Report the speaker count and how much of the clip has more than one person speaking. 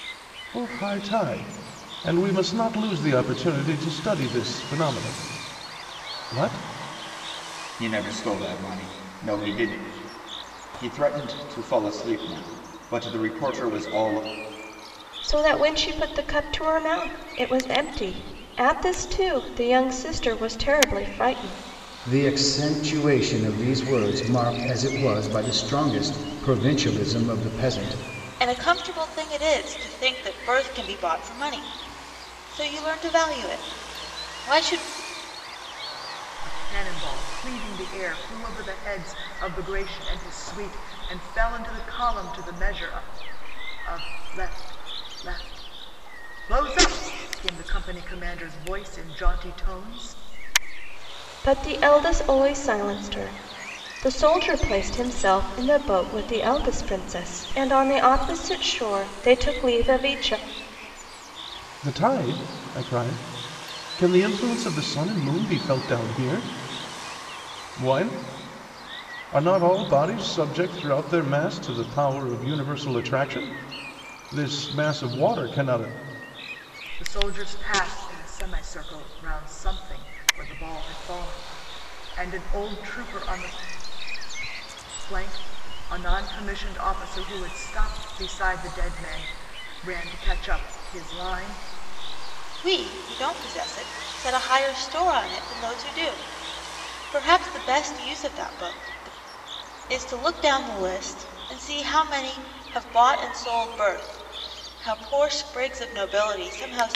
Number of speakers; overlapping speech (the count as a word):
six, no overlap